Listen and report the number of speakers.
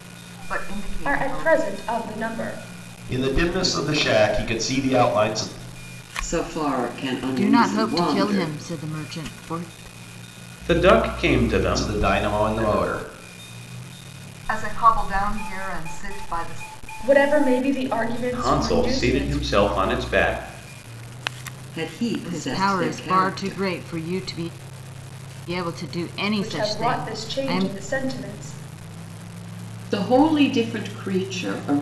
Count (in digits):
6